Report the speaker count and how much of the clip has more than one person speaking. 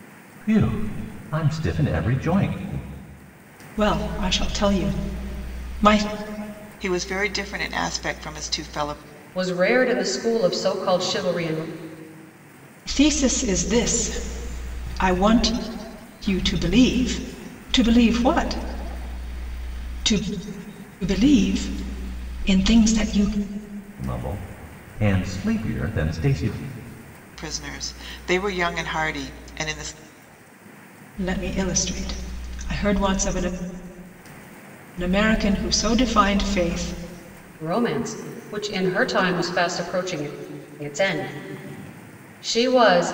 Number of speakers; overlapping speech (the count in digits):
4, no overlap